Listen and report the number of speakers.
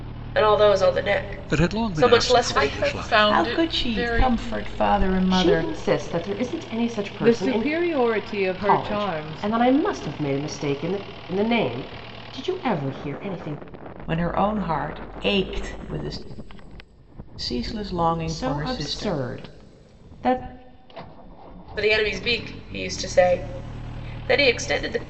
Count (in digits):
6